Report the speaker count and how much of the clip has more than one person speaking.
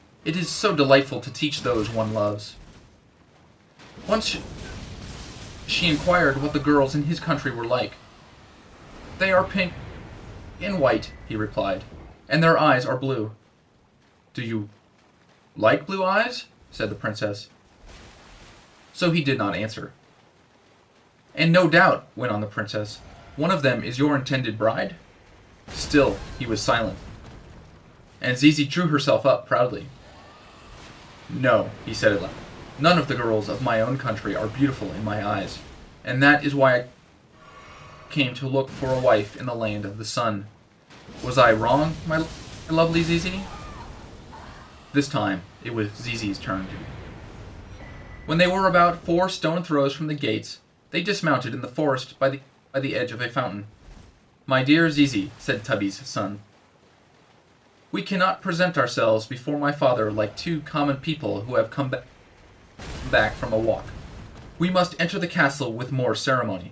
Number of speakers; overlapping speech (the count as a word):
one, no overlap